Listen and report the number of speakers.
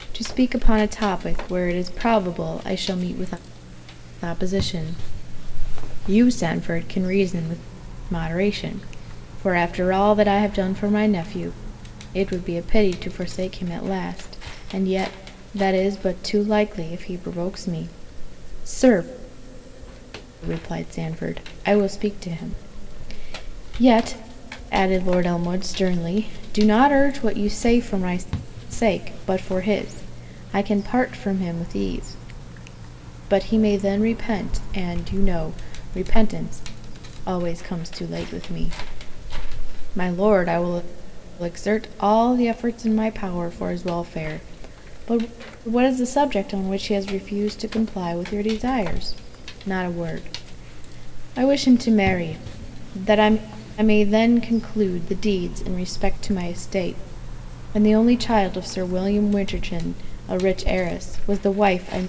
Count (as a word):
one